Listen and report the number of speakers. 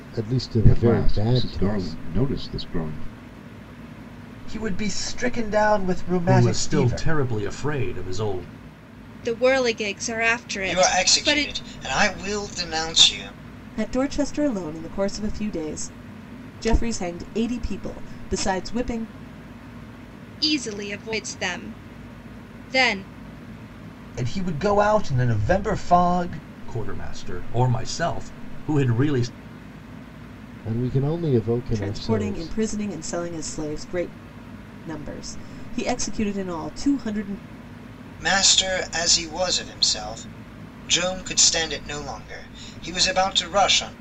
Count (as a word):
seven